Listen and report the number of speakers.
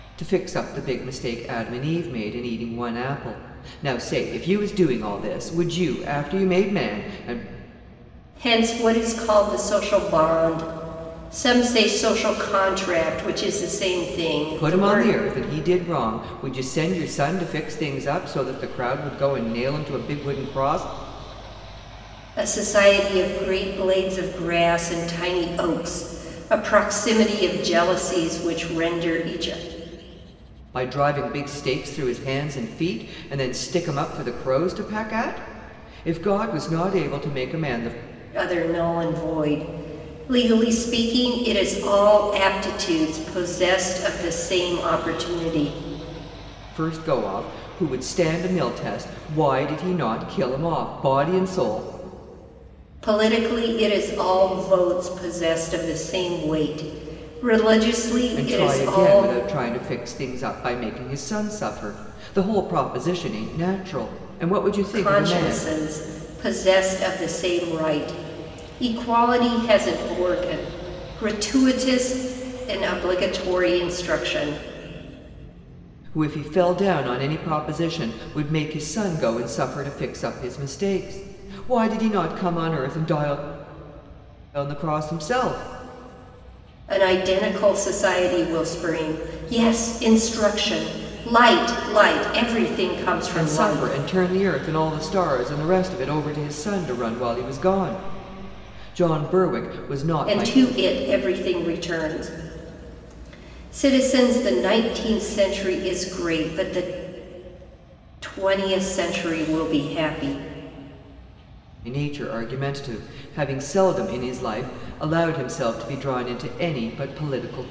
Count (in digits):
2